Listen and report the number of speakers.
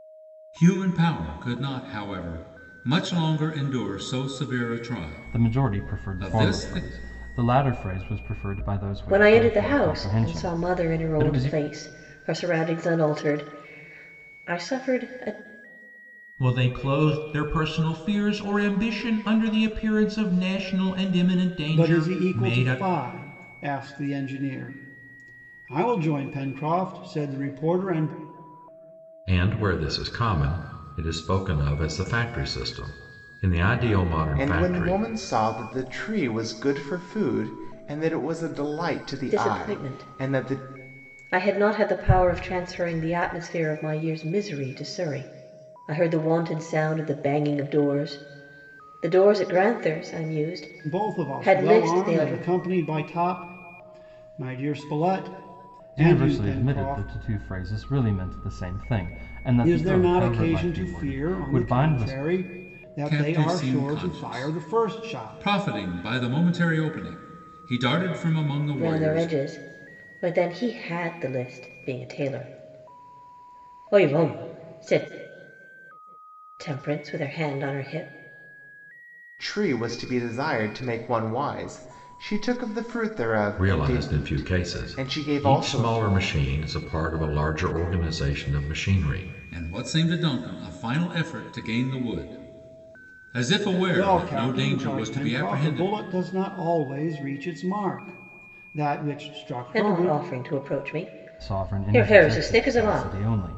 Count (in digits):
7